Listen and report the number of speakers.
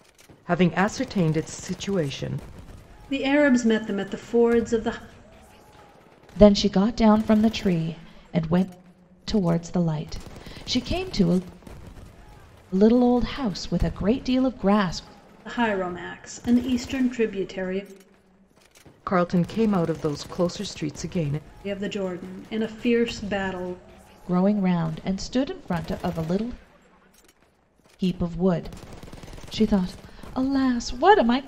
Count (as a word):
three